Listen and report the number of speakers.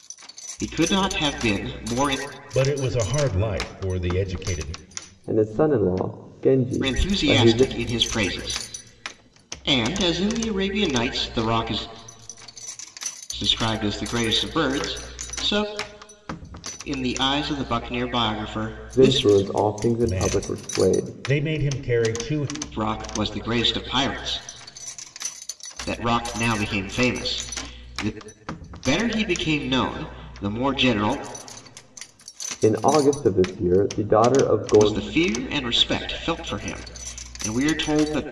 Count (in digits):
3